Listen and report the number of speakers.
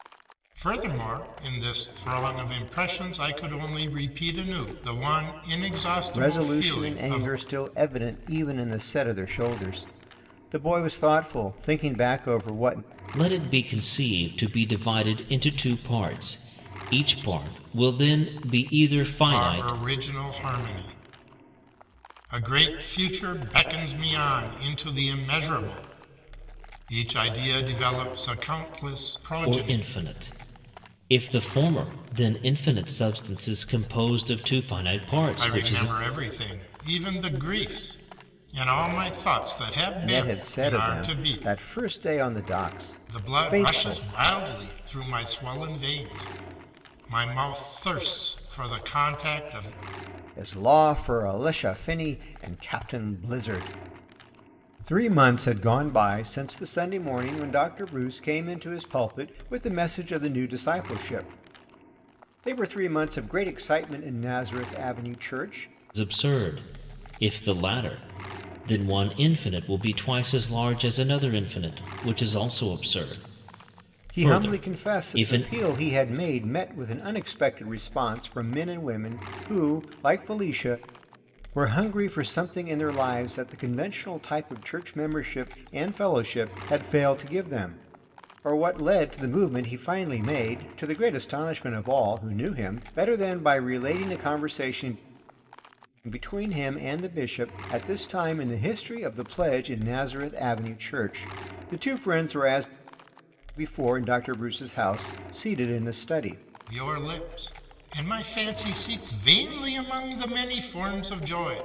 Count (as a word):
three